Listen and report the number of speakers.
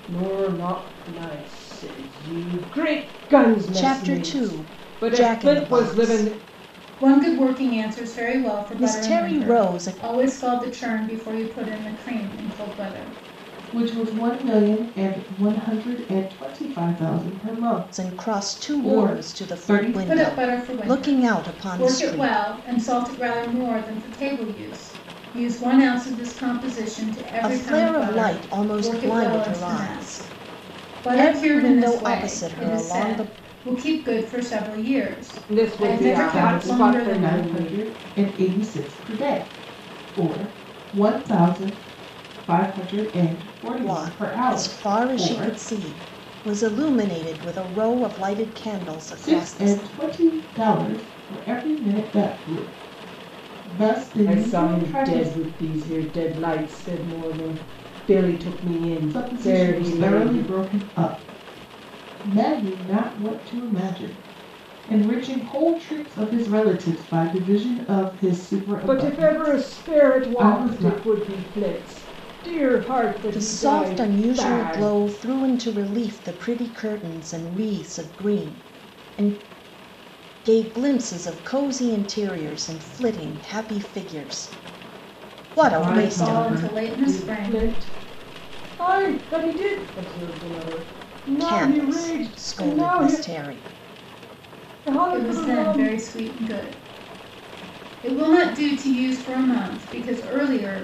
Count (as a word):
four